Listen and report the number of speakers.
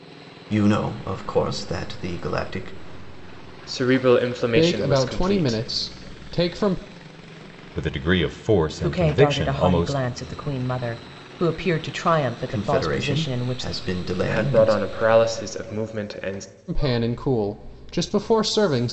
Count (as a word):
five